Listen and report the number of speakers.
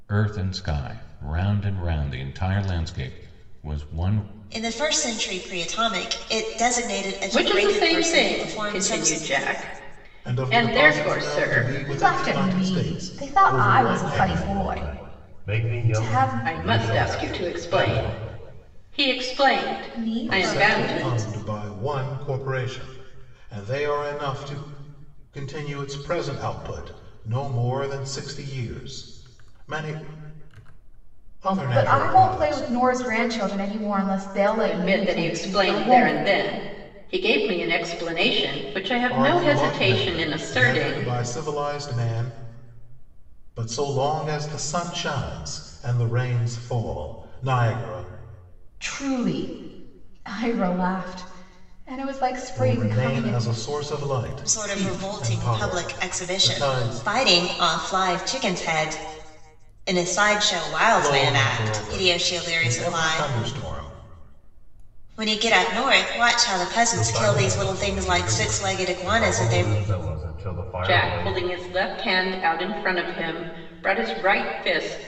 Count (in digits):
6